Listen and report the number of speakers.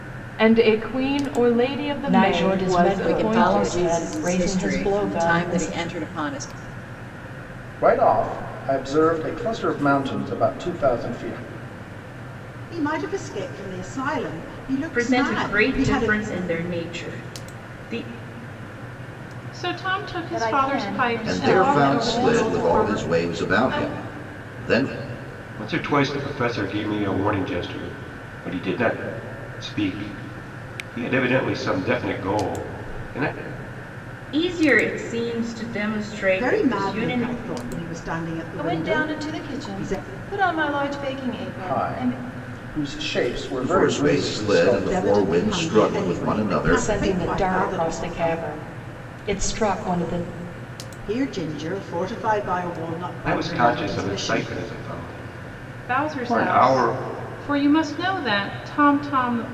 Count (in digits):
10